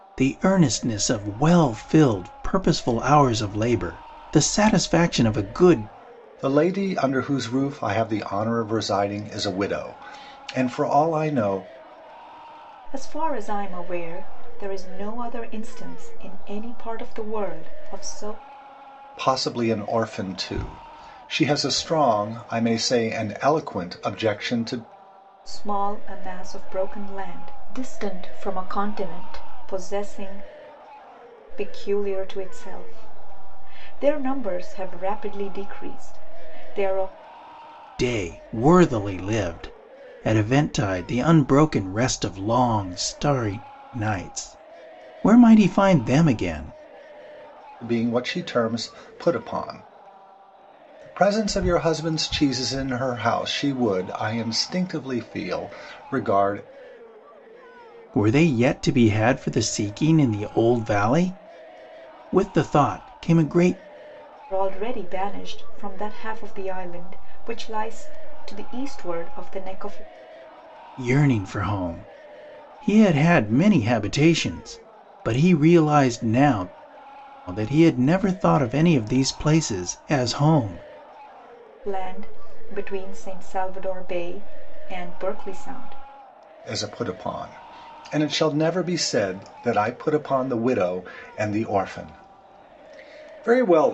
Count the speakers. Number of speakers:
three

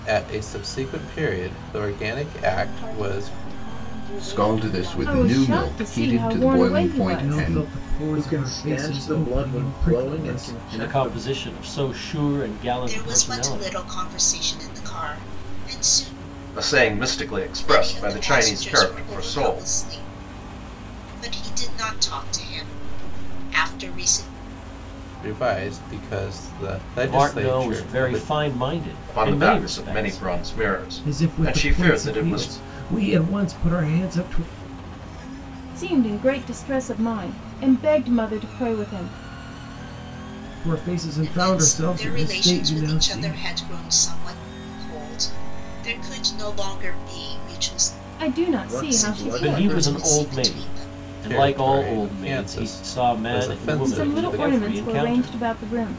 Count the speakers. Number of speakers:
nine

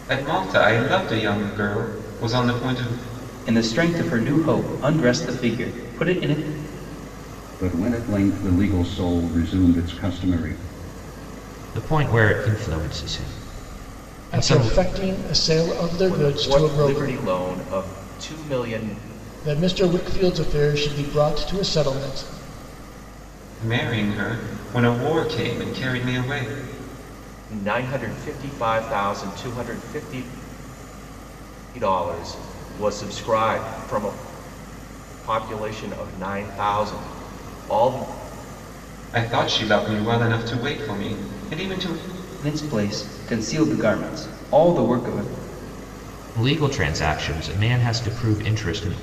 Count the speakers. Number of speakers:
six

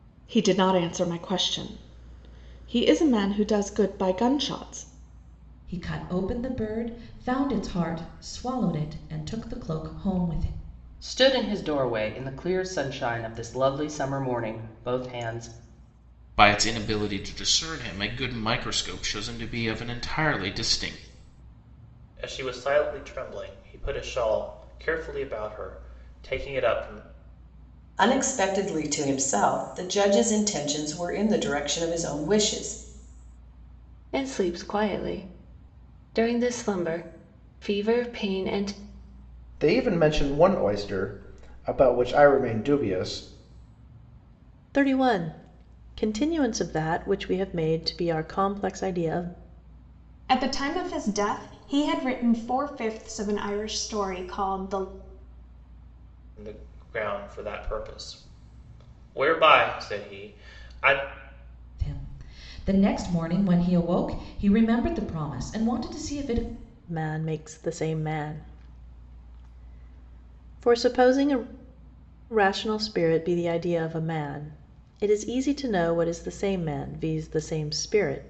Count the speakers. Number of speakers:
ten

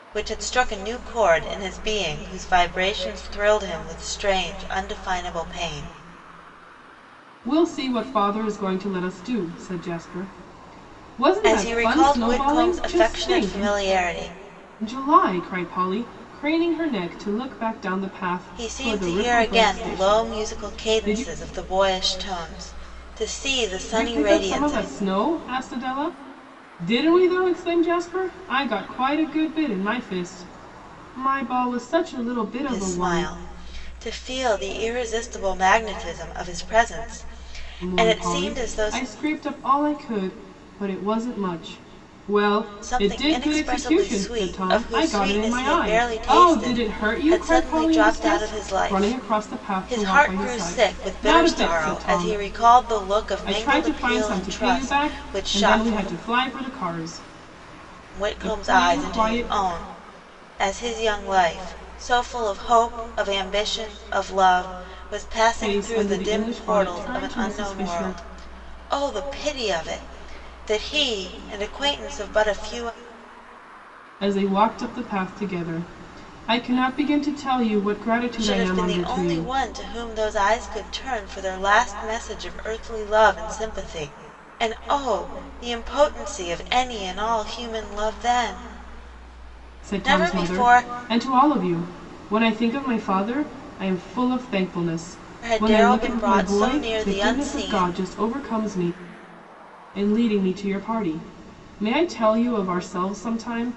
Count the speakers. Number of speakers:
two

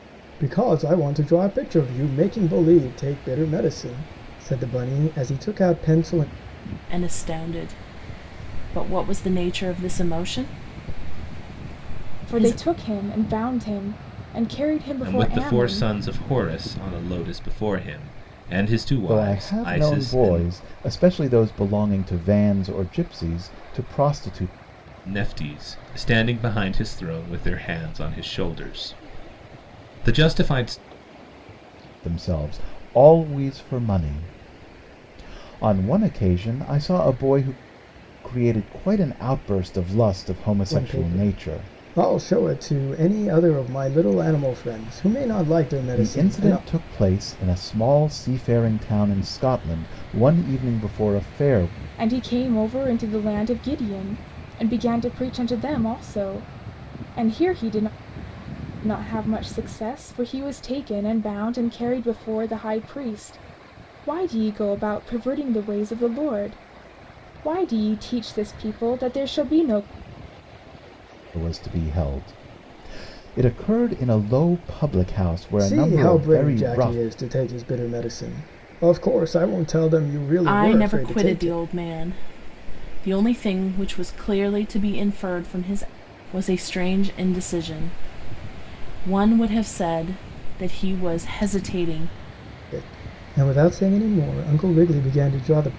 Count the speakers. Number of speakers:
five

